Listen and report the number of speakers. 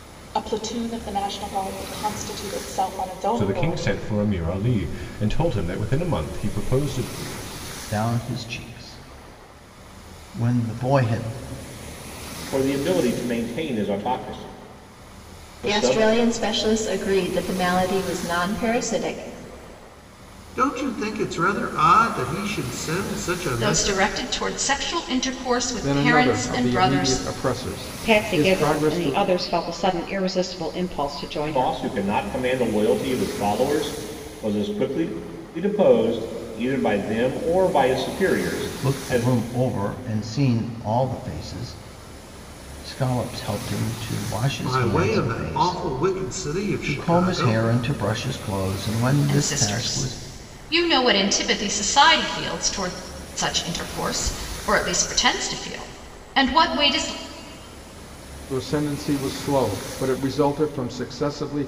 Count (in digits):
9